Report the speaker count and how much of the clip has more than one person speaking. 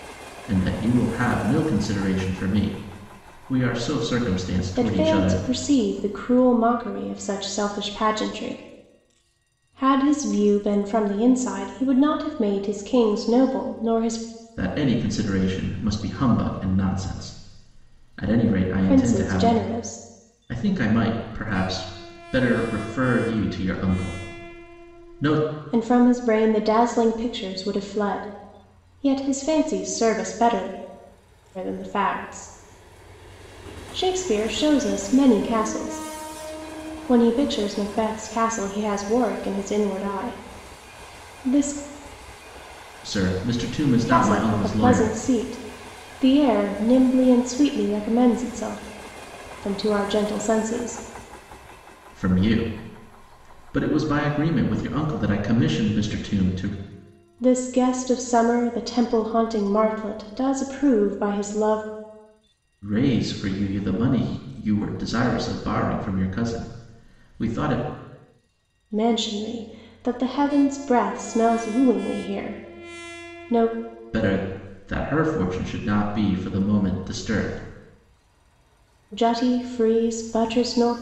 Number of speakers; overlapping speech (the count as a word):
two, about 3%